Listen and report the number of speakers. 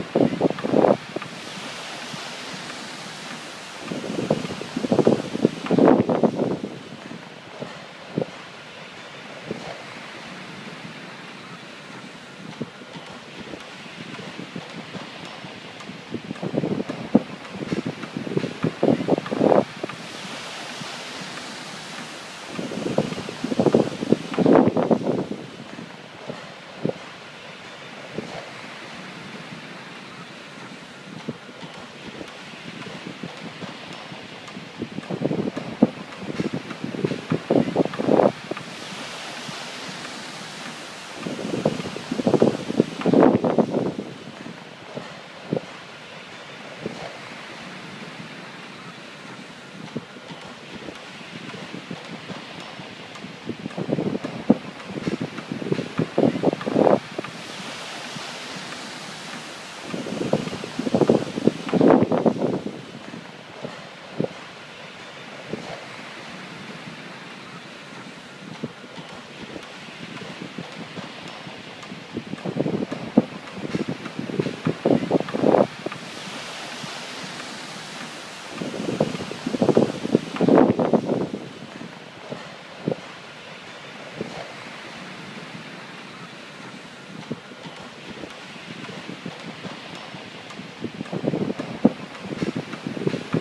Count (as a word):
zero